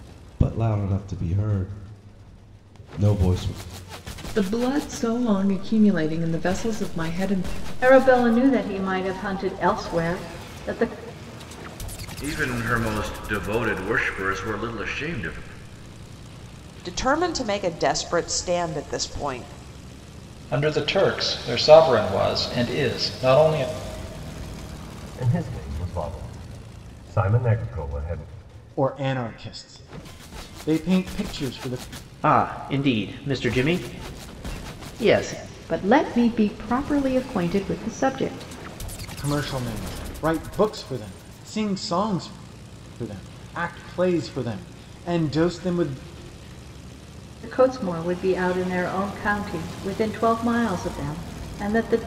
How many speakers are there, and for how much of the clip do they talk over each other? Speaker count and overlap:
10, no overlap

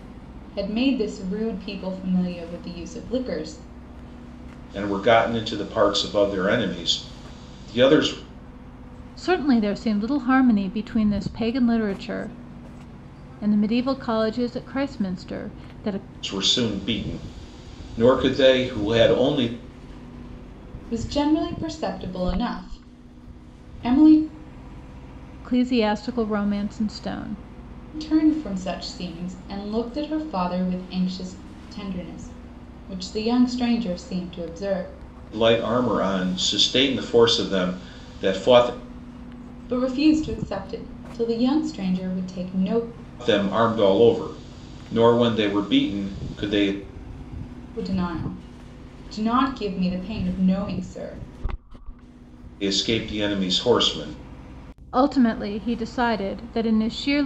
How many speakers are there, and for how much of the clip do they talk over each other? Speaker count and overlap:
3, no overlap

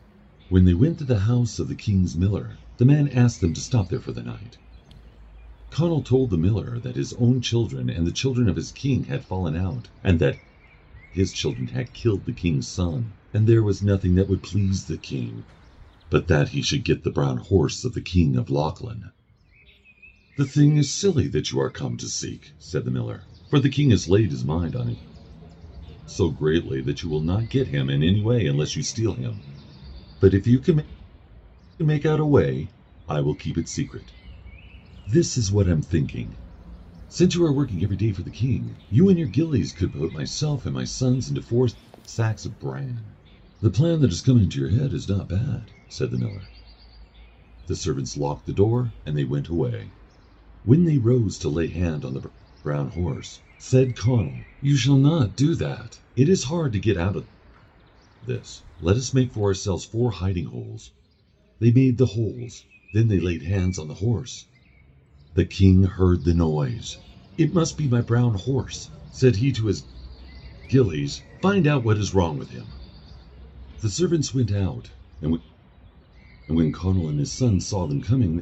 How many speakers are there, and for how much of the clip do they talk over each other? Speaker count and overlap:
1, no overlap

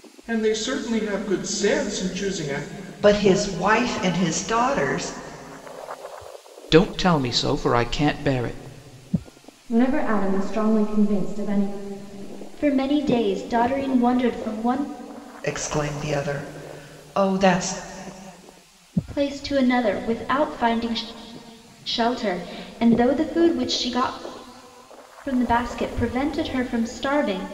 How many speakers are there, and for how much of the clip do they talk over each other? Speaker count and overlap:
5, no overlap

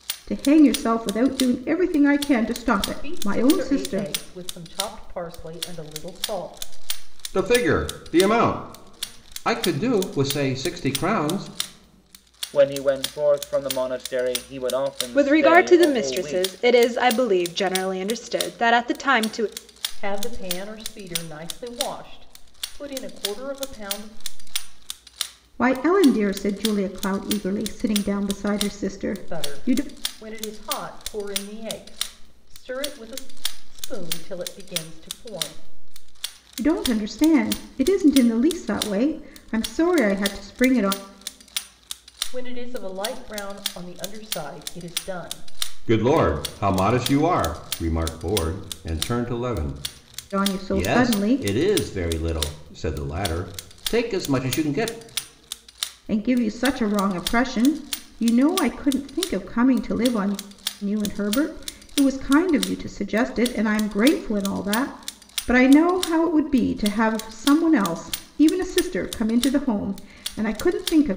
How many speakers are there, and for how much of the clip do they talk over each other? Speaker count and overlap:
5, about 6%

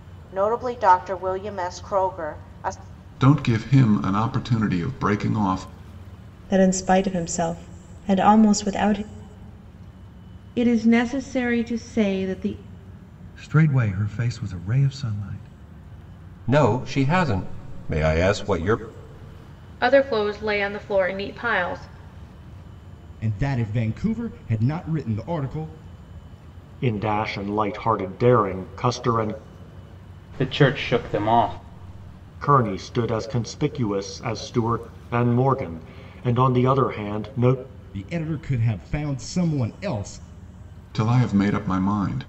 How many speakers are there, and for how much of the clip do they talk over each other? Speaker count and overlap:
10, no overlap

